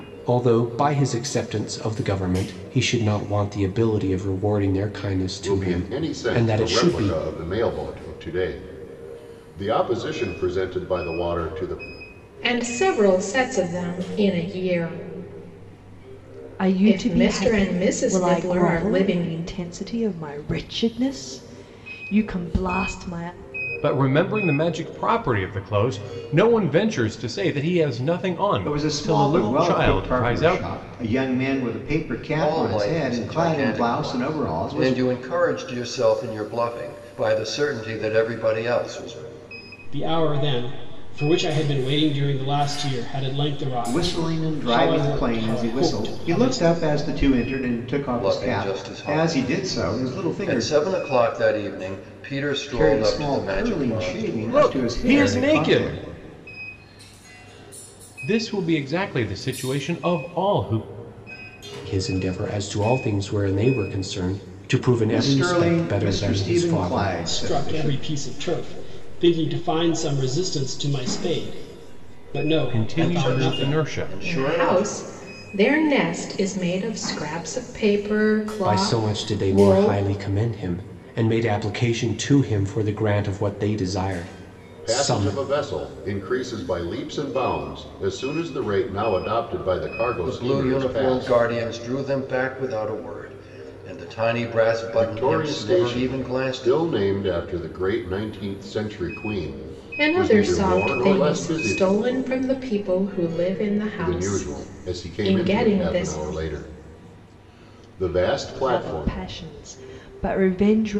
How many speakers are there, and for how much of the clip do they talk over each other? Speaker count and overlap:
eight, about 30%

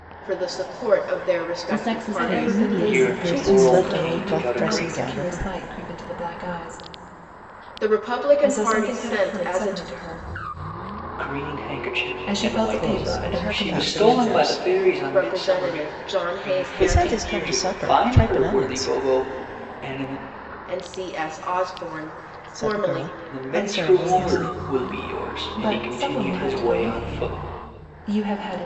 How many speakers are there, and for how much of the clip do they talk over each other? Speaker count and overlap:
five, about 56%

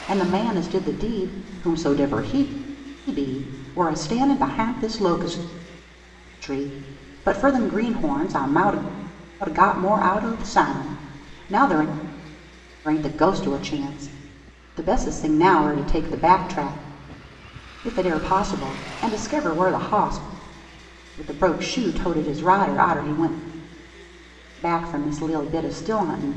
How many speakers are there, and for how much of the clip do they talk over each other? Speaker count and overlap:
one, no overlap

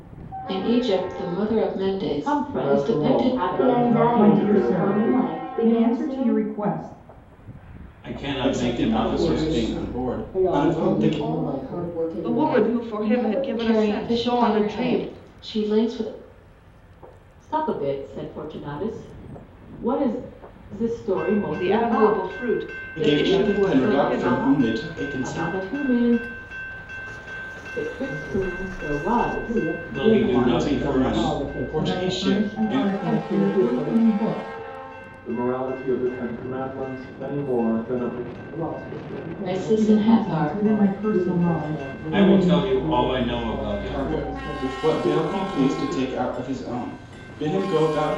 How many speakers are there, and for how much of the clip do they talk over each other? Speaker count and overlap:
ten, about 56%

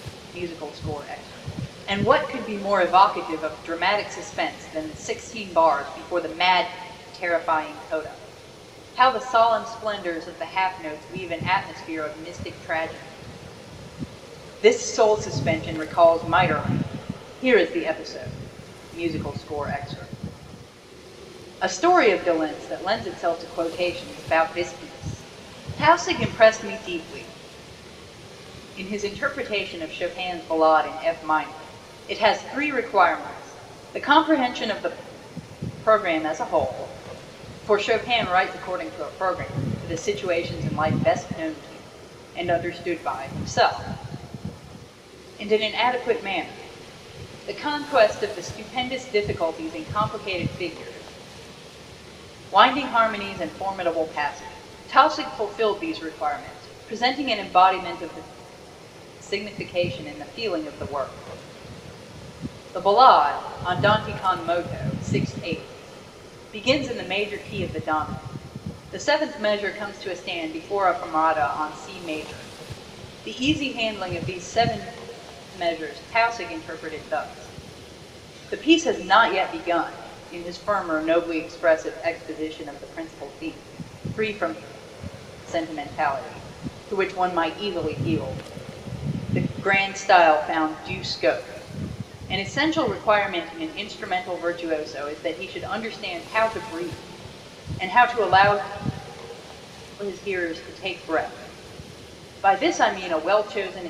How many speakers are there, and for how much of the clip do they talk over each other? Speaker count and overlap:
one, no overlap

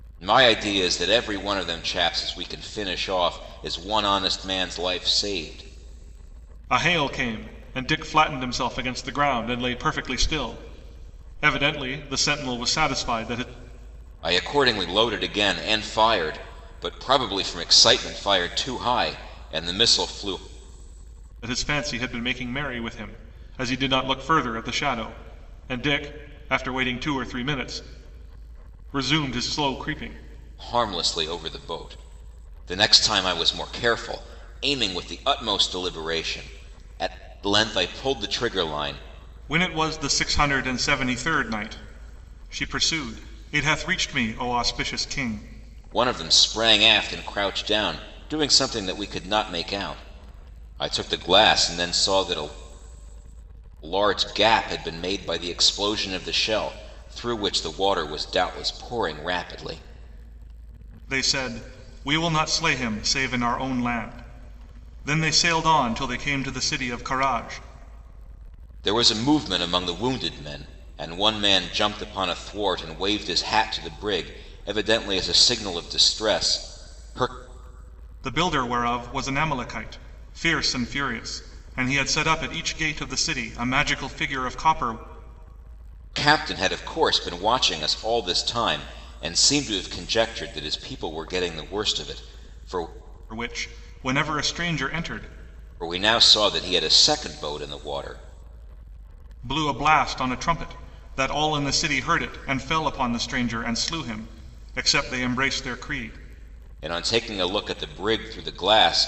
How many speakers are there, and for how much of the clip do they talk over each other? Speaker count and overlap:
two, no overlap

